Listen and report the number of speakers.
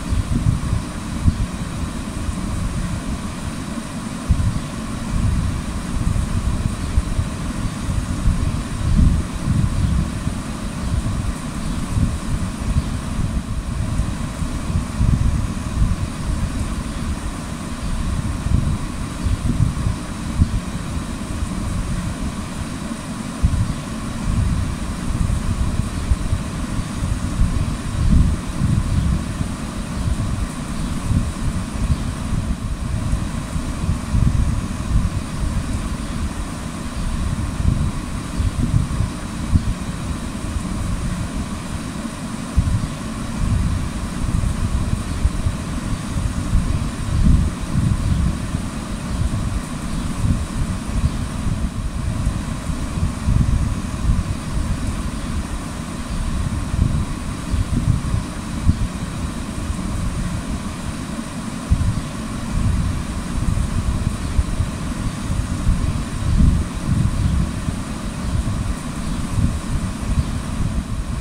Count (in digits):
0